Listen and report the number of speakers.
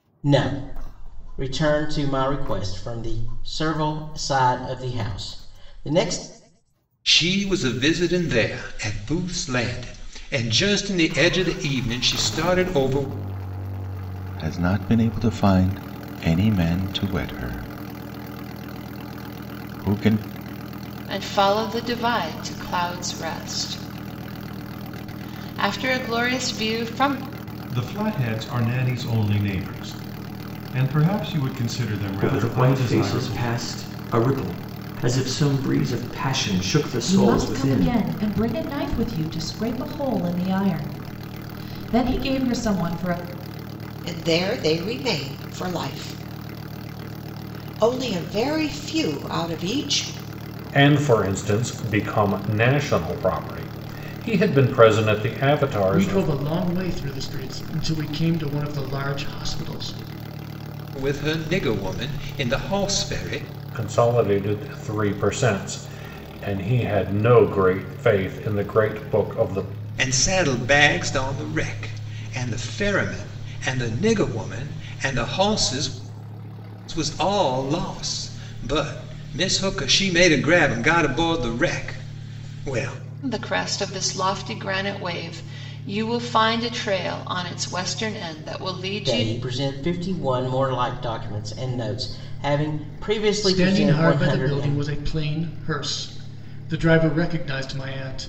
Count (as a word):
ten